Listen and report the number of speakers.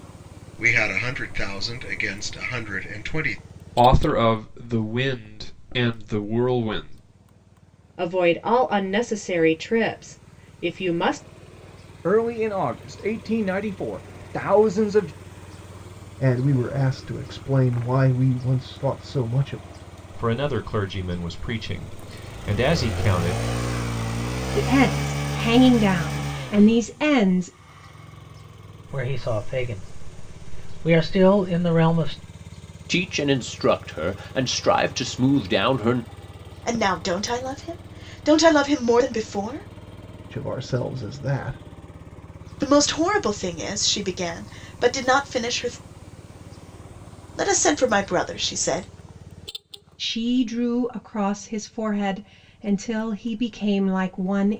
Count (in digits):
10